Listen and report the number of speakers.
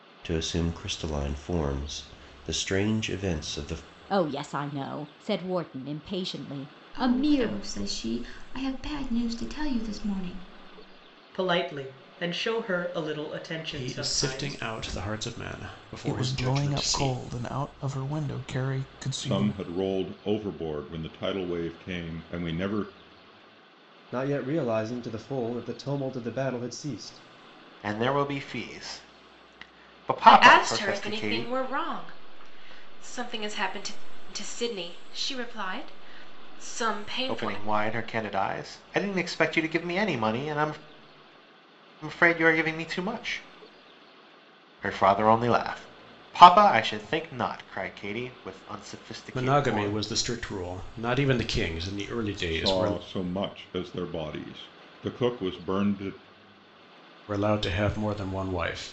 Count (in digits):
10